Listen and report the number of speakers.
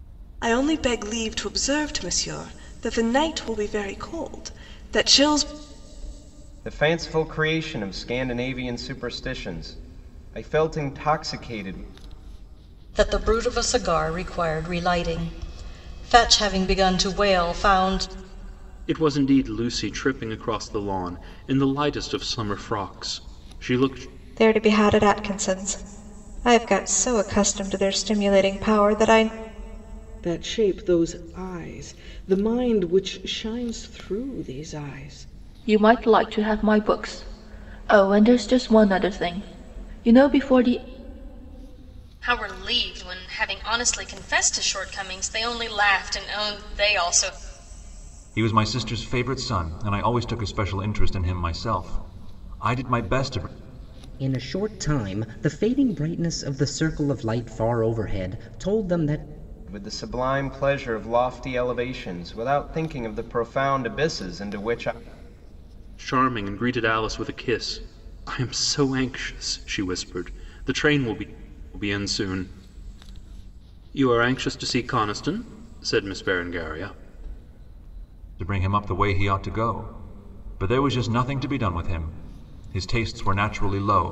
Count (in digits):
10